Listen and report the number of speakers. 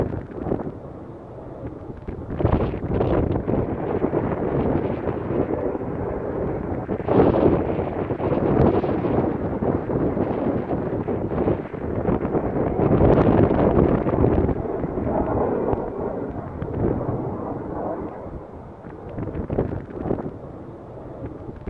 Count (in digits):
0